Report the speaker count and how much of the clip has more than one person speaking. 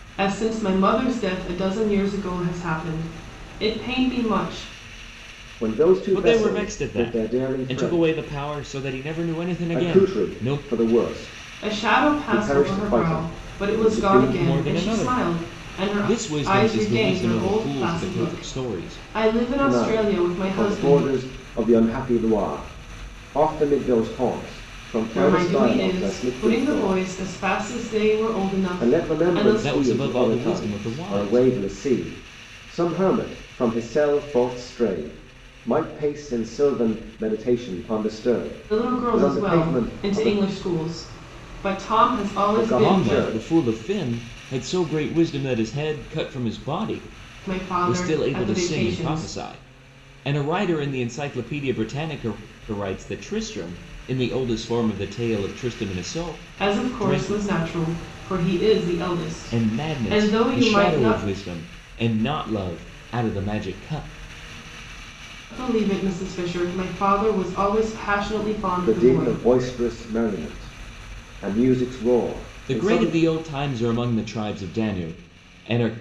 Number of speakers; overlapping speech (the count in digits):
3, about 32%